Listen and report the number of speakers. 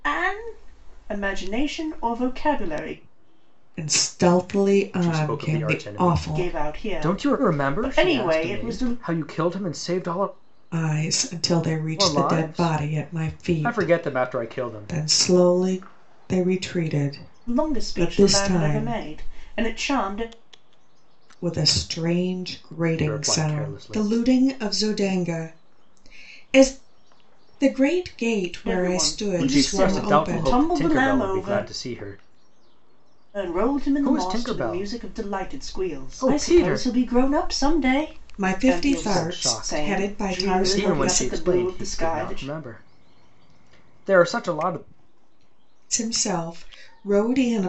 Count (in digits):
3